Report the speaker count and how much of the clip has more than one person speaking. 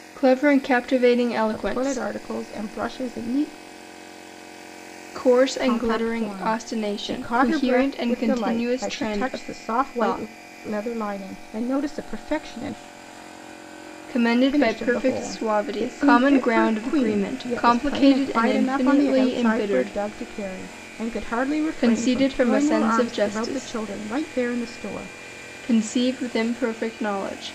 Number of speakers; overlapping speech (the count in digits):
2, about 46%